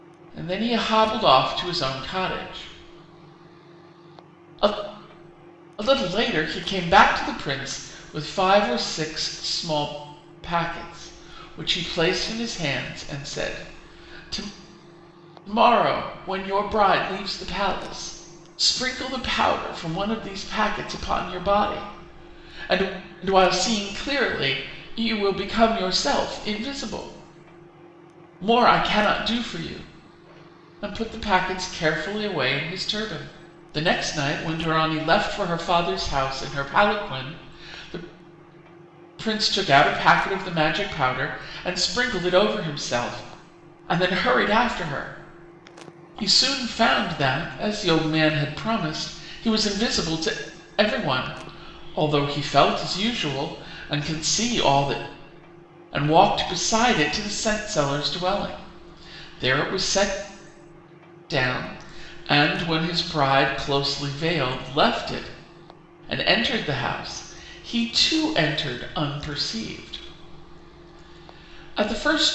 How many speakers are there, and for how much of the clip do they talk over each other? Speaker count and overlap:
1, no overlap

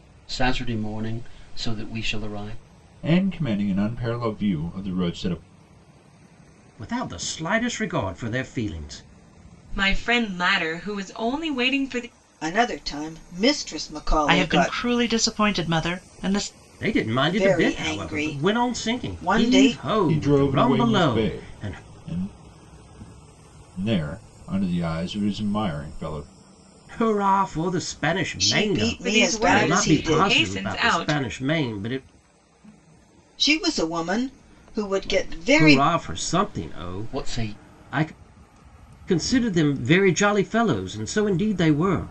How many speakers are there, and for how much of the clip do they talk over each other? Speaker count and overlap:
6, about 24%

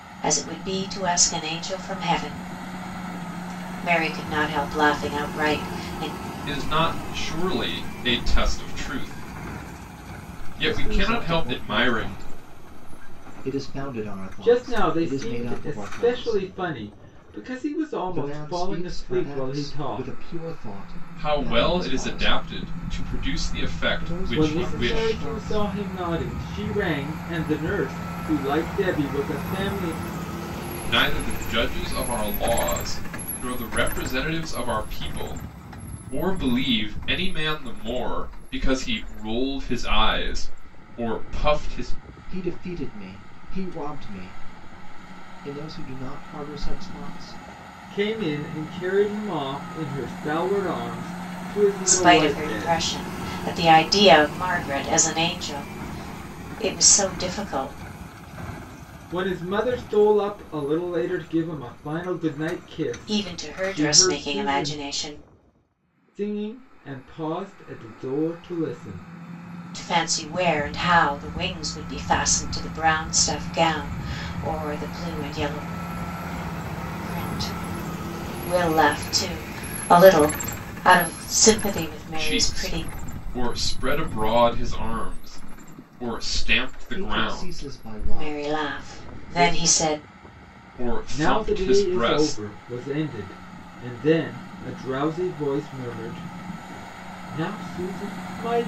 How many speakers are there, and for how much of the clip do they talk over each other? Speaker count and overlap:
4, about 16%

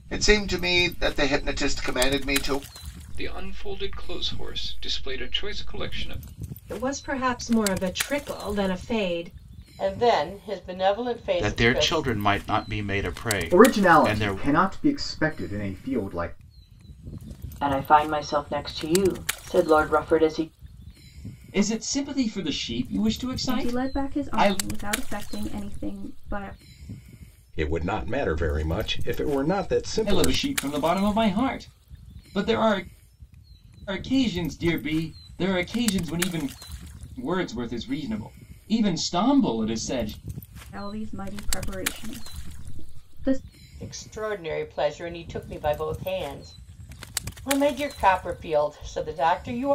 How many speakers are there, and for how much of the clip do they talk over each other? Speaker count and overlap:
10, about 6%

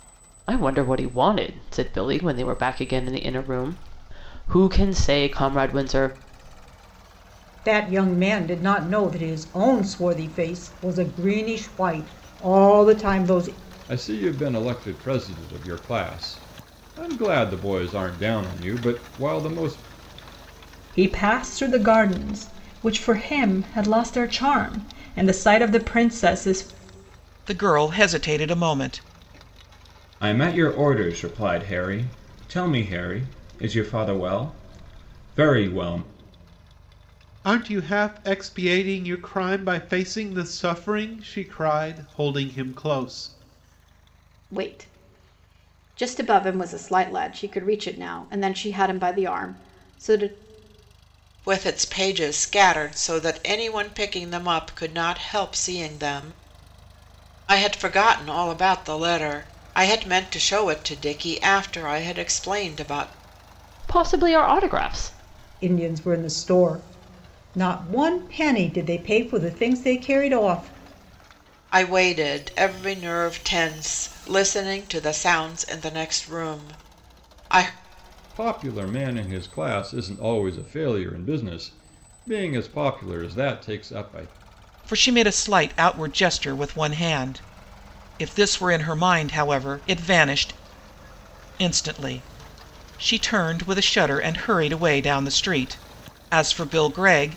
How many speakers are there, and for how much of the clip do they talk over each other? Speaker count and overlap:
9, no overlap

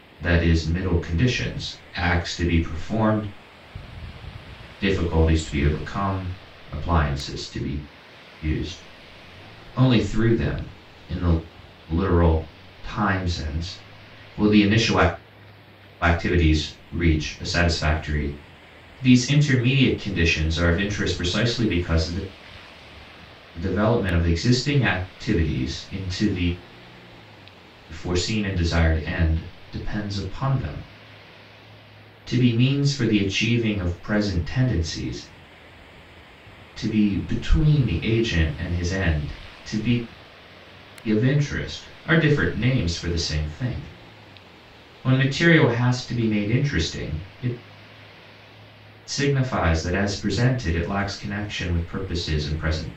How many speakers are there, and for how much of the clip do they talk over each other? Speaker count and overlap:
1, no overlap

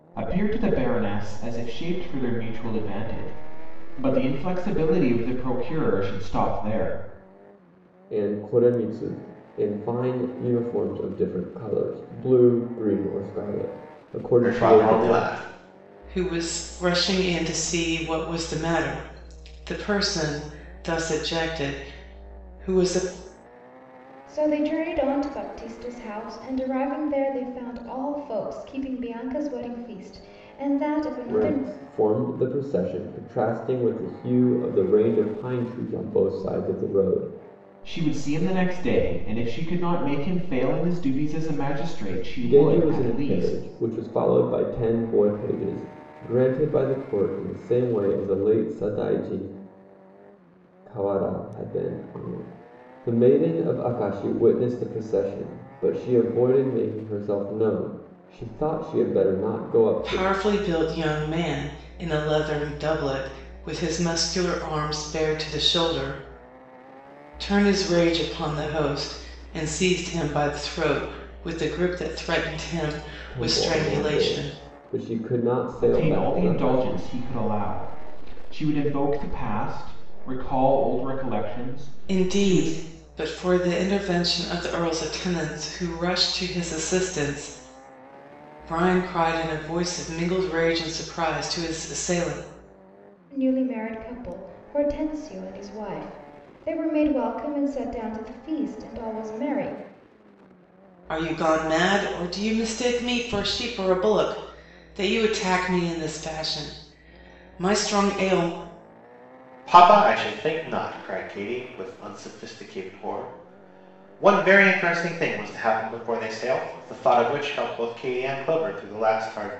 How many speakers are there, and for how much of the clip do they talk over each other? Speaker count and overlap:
5, about 5%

